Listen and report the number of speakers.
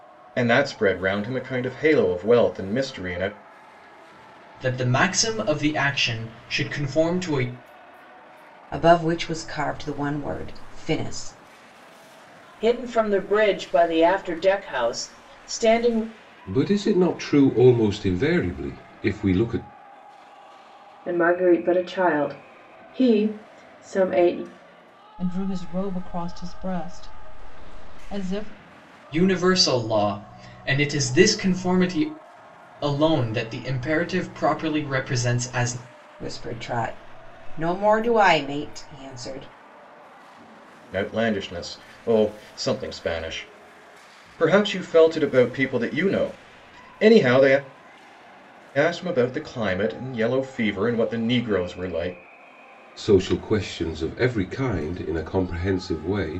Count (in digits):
7